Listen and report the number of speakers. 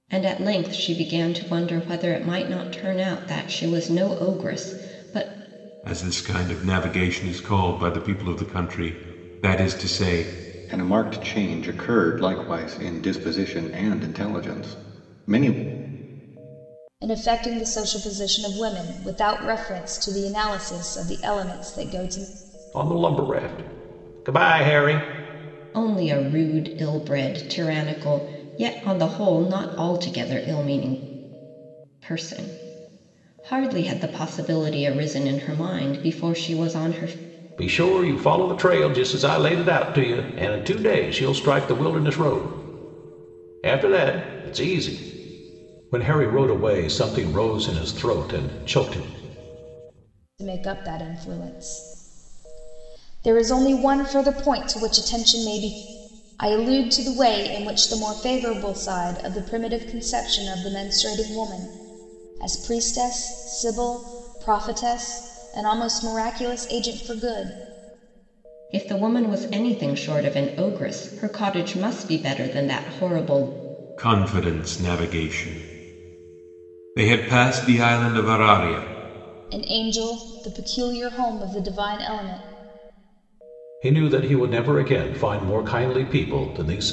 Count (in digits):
5